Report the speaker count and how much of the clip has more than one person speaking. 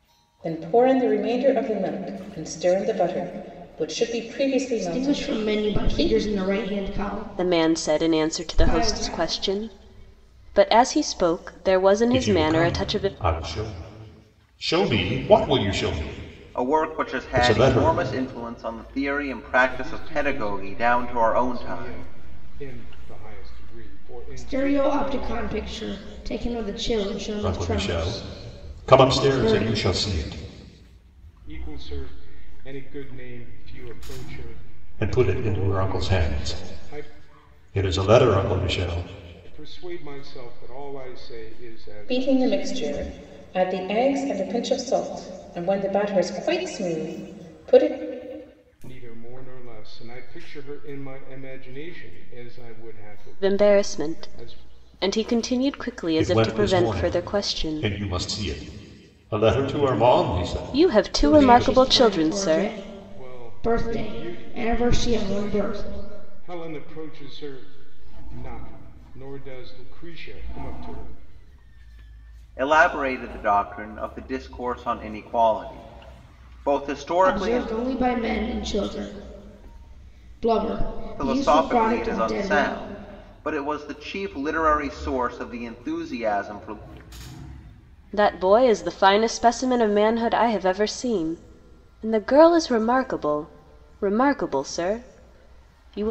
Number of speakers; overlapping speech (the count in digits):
6, about 27%